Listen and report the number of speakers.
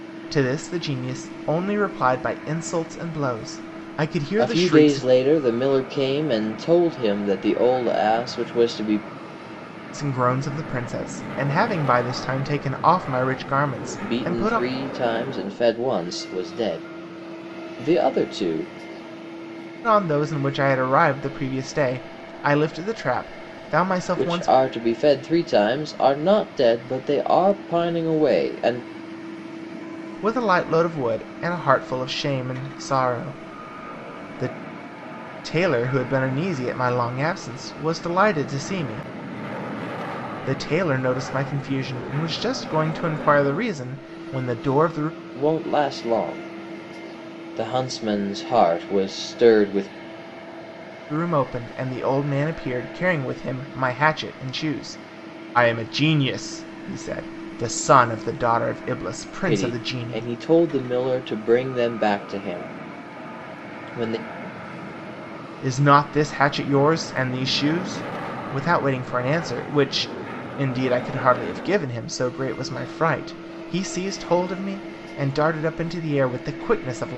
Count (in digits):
2